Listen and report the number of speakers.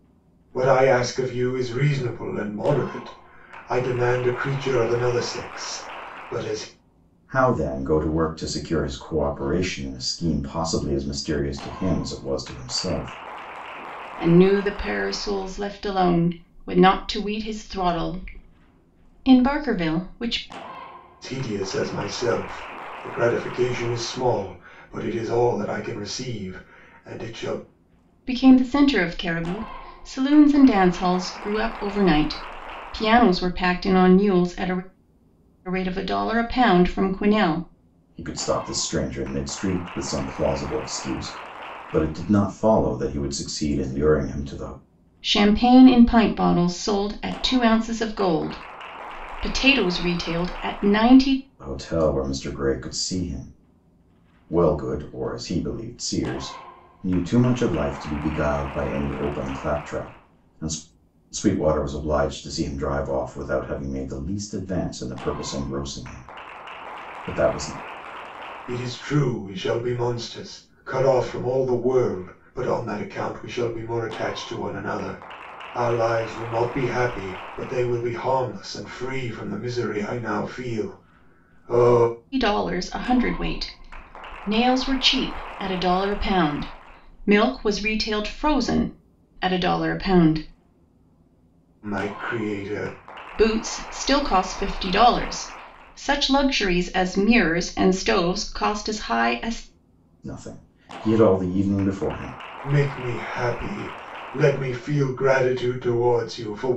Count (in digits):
3